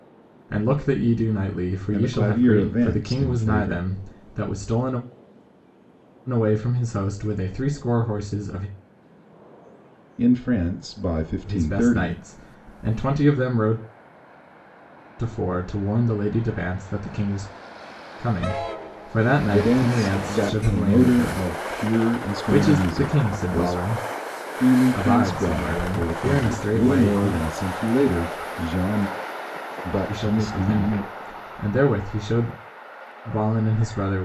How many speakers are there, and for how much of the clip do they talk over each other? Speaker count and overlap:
two, about 30%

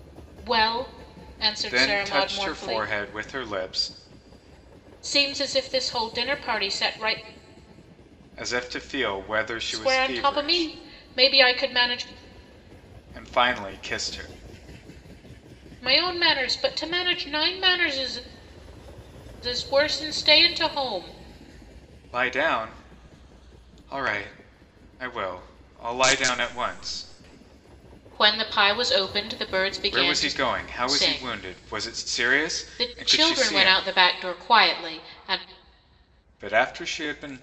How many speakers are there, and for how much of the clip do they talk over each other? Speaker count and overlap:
two, about 15%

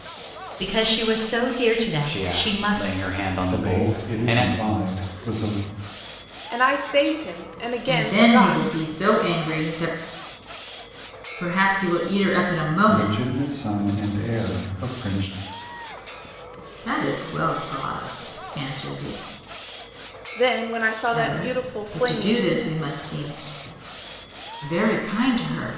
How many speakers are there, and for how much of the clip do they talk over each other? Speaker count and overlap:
five, about 18%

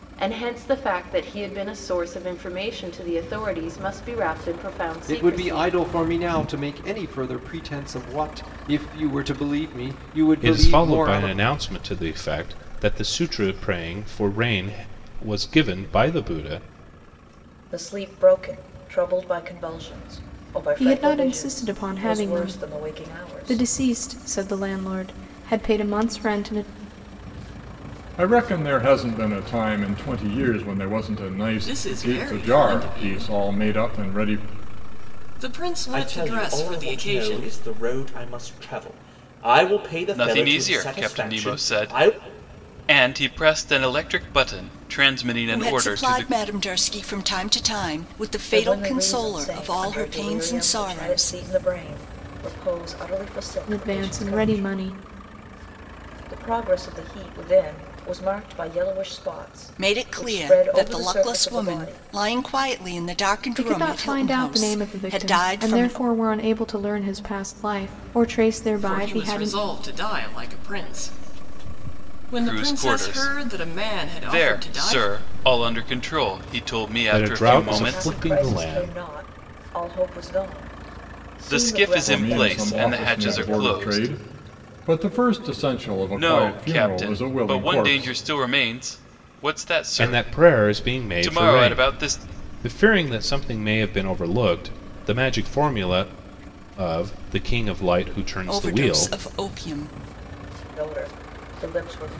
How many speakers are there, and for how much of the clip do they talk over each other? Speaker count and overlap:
ten, about 33%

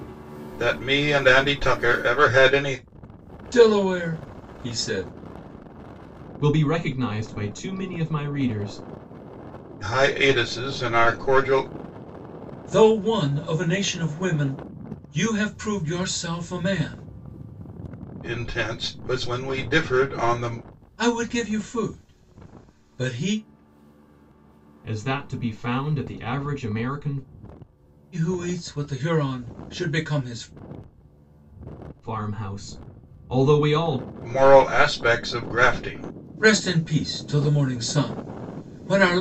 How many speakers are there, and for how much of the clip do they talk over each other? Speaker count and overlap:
three, no overlap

